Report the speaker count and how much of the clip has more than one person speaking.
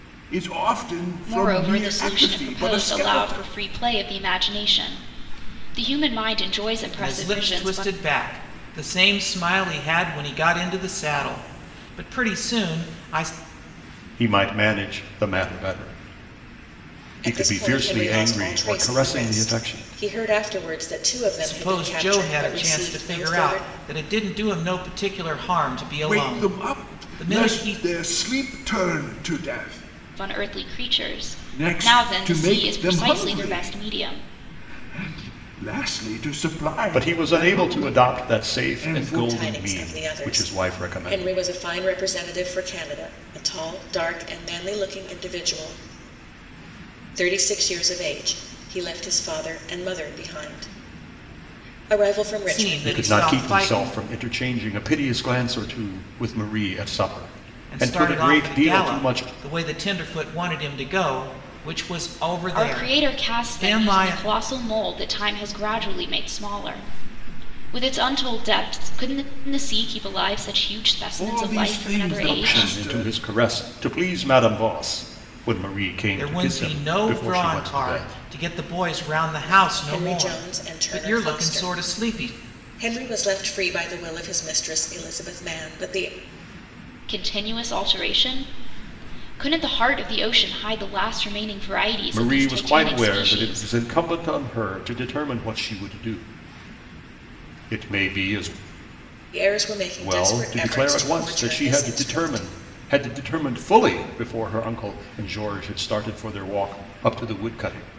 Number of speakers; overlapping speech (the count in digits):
5, about 32%